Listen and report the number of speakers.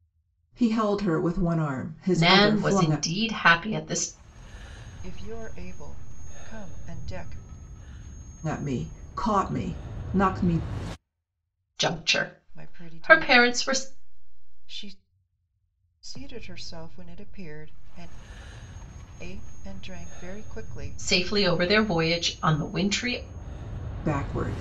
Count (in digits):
3